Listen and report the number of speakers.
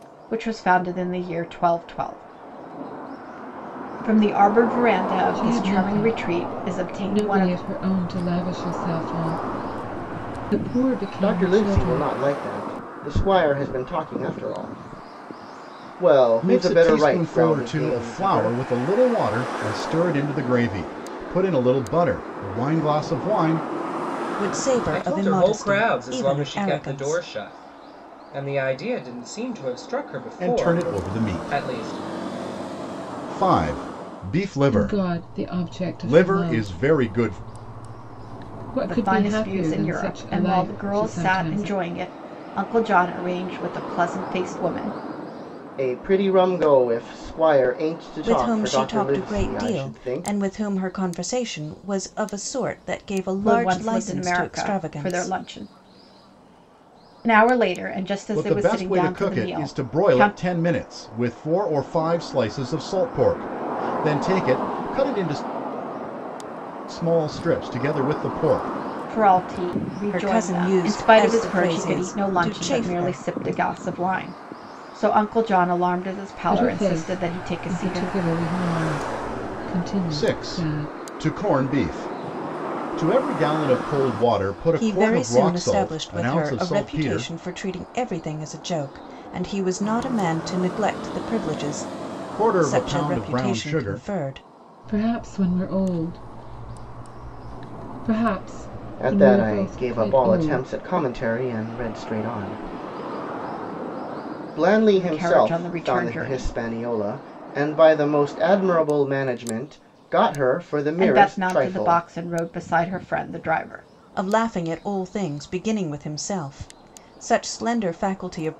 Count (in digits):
6